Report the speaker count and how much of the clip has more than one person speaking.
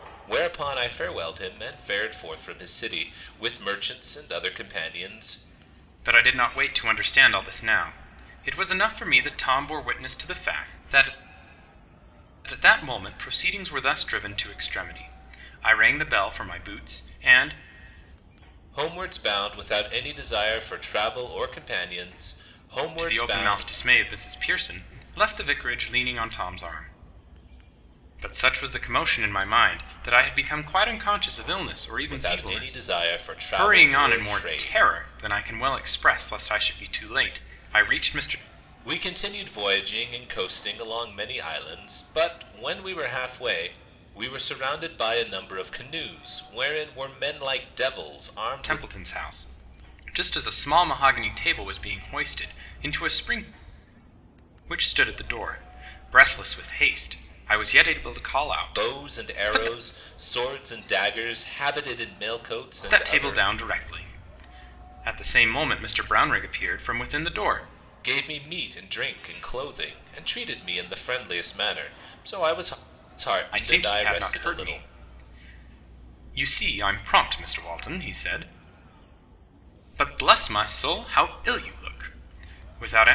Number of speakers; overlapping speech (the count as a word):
two, about 8%